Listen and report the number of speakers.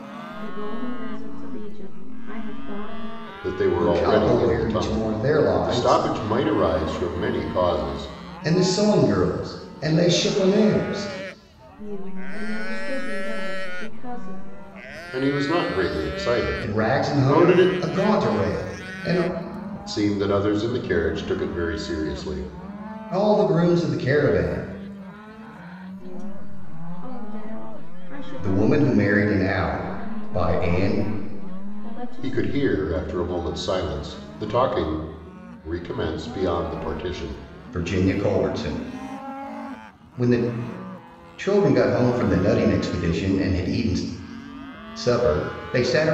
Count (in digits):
3